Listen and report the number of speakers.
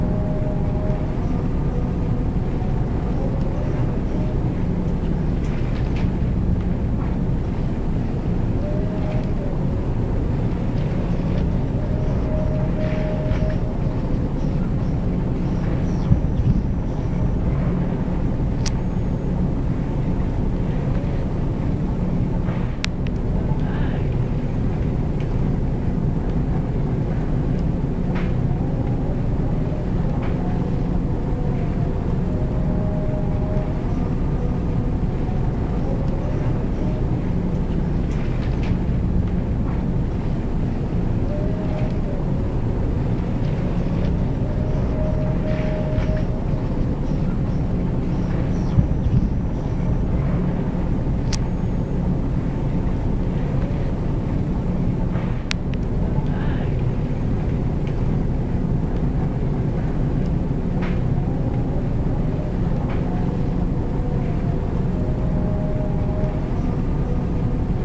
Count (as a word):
zero